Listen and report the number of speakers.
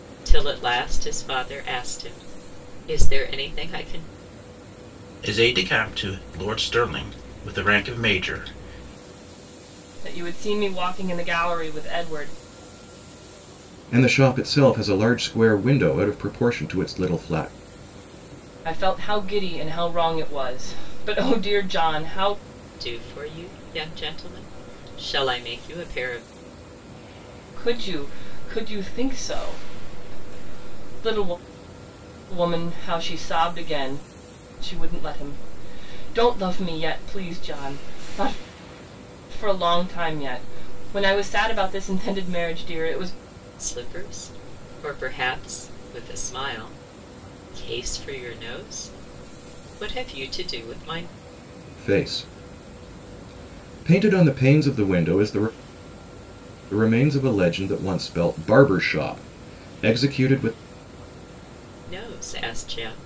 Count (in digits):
4